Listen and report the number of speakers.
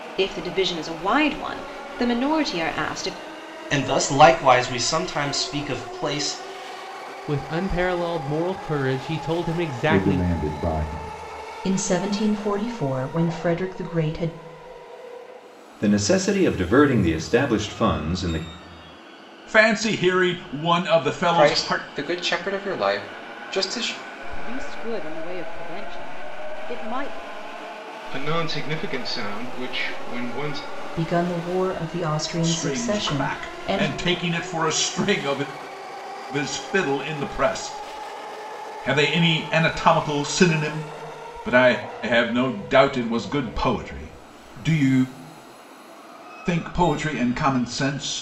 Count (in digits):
10